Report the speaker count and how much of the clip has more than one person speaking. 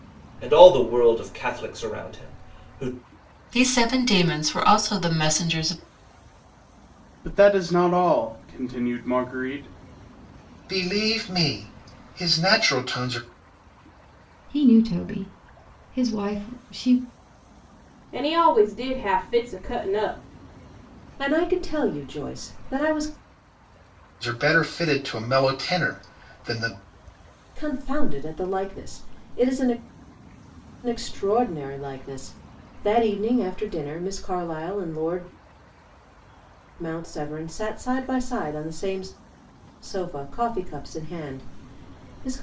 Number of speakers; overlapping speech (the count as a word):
seven, no overlap